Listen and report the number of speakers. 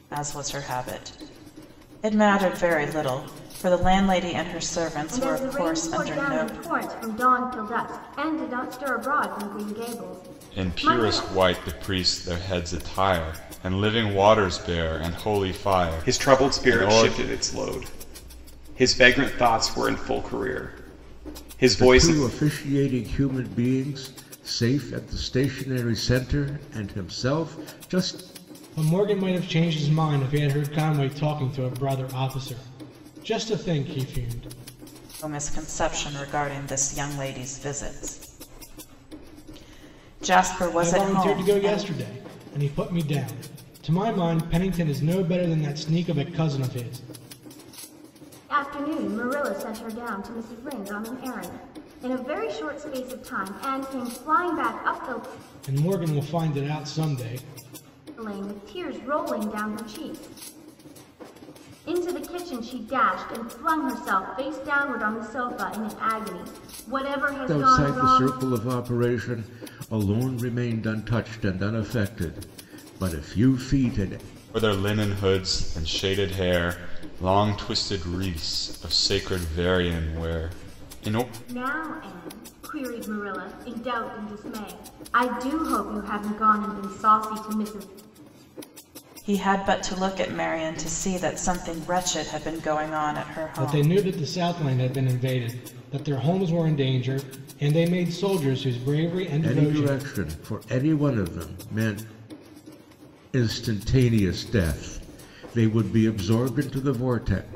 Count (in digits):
6